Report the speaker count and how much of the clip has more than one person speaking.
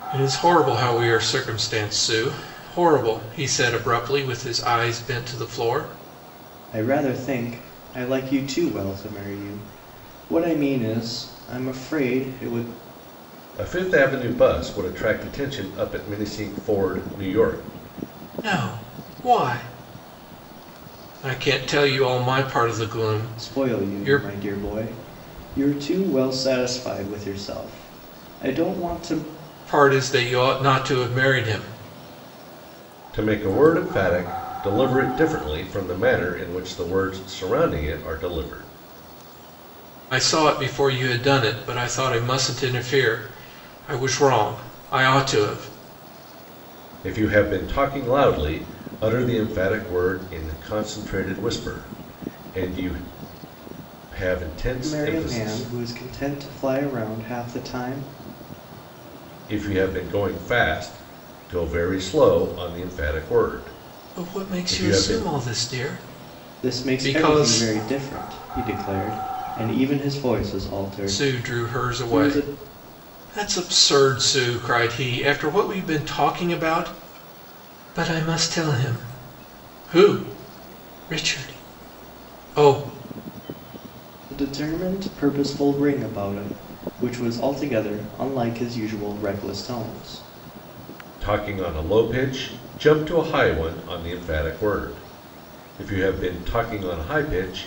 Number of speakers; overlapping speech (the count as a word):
three, about 6%